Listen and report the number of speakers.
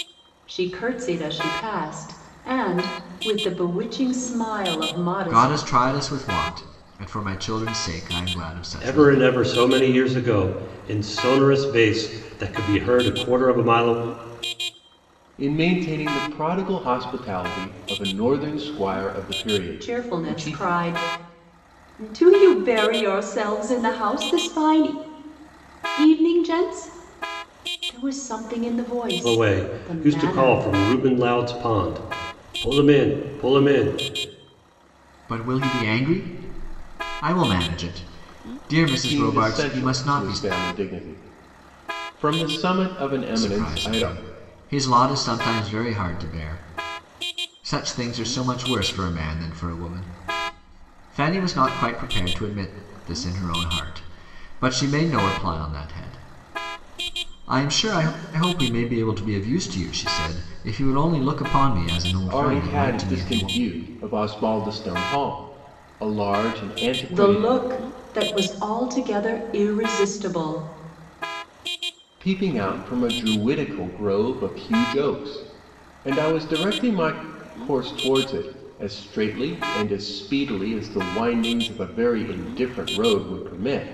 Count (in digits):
4